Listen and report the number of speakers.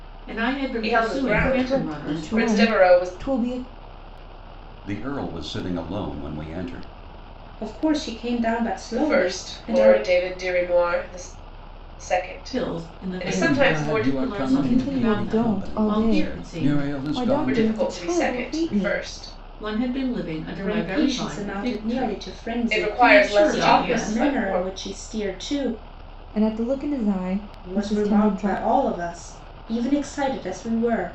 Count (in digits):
5